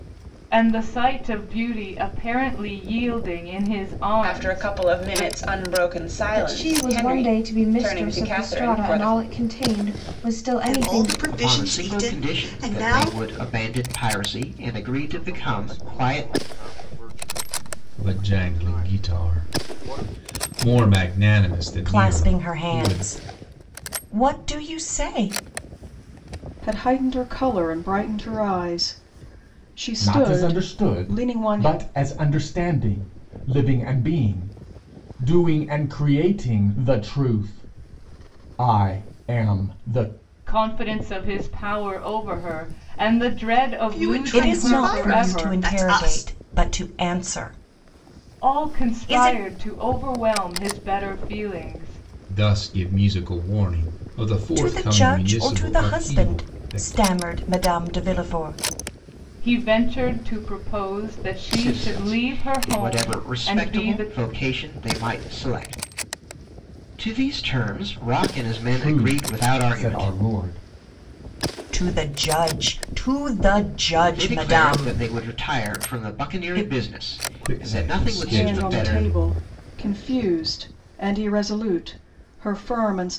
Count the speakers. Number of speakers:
10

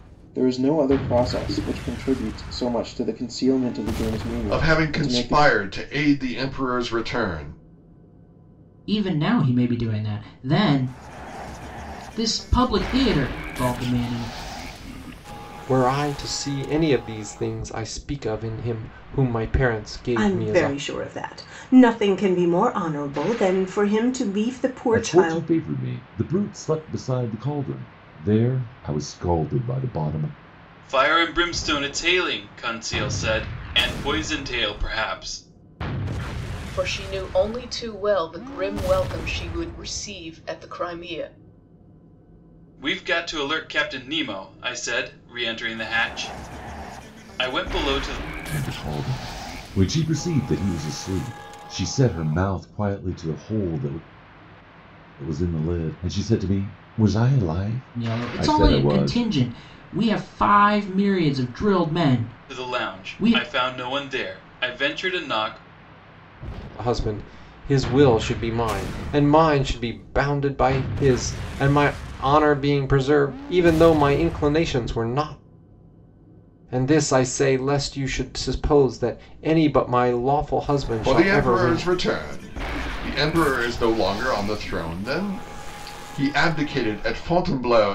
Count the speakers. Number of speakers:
8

